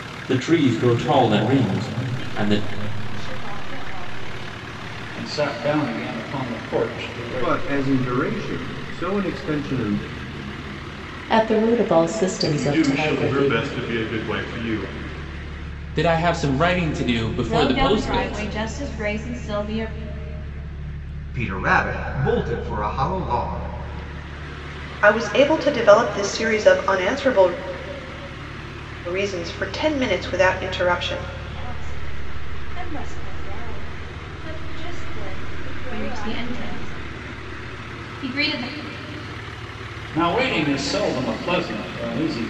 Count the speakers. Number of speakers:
10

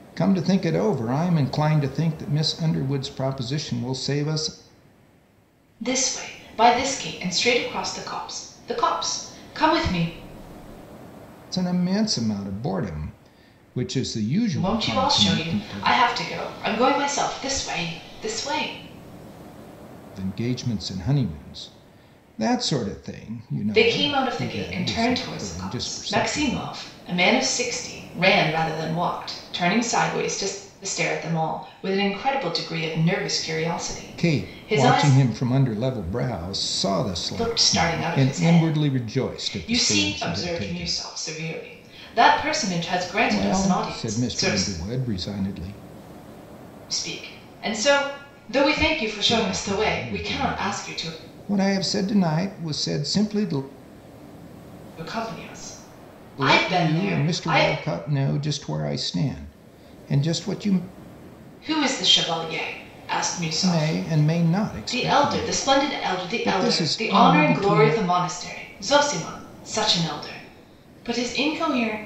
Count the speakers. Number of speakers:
2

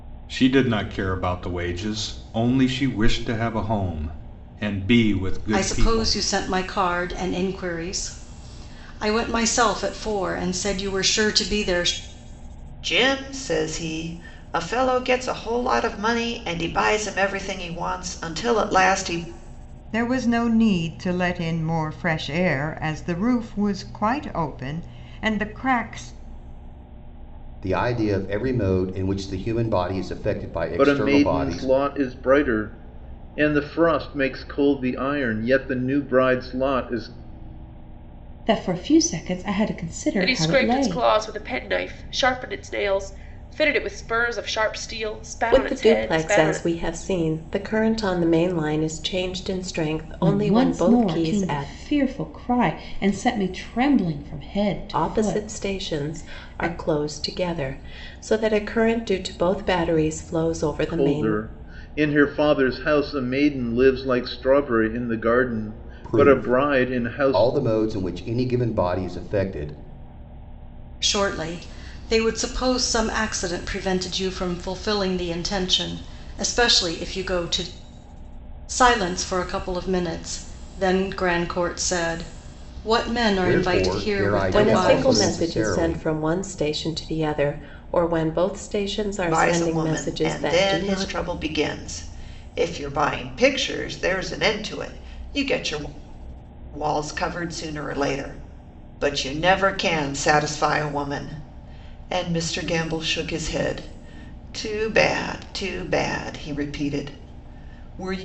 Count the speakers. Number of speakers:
9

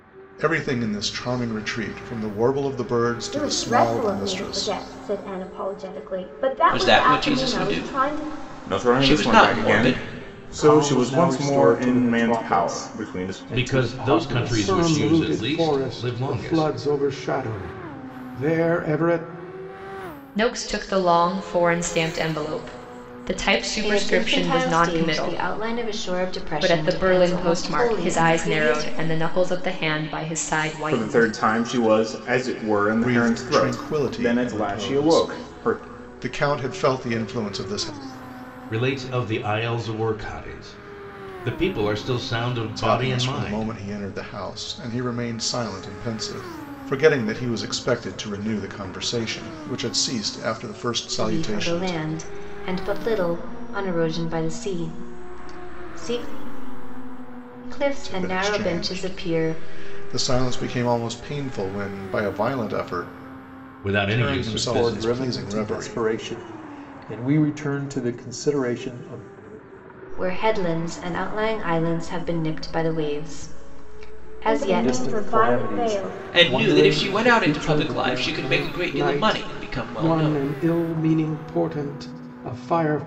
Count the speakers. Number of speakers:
9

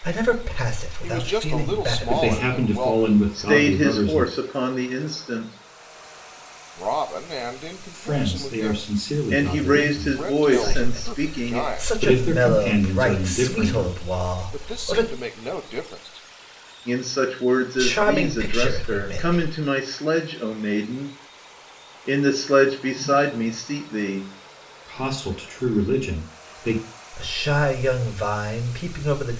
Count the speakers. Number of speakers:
4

